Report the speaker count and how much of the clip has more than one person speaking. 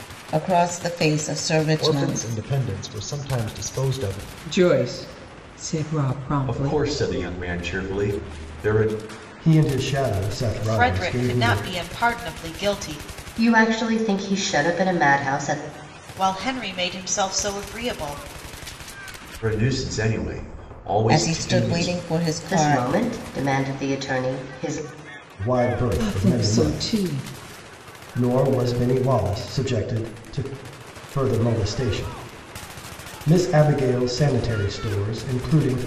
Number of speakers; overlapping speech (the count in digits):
7, about 12%